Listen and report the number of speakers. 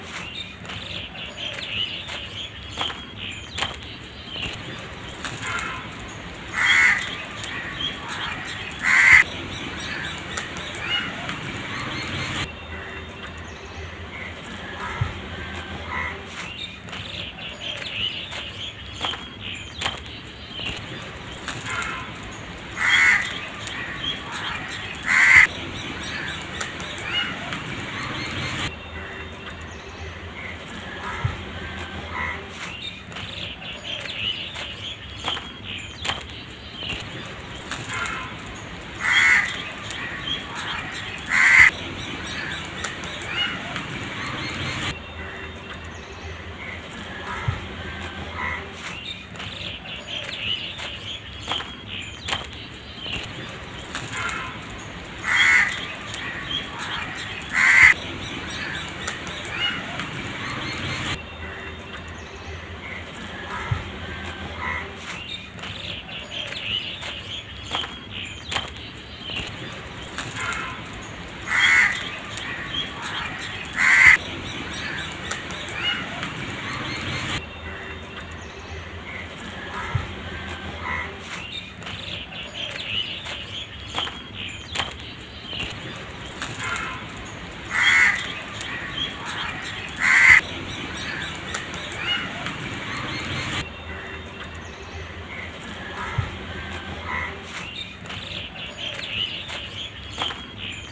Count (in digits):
0